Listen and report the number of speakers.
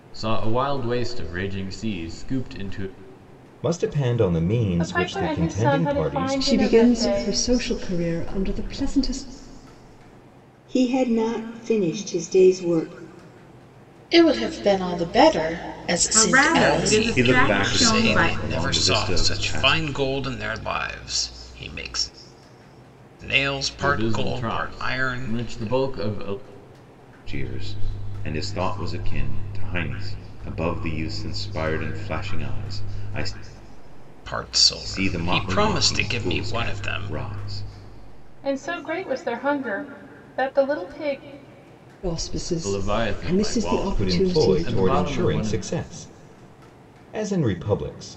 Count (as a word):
nine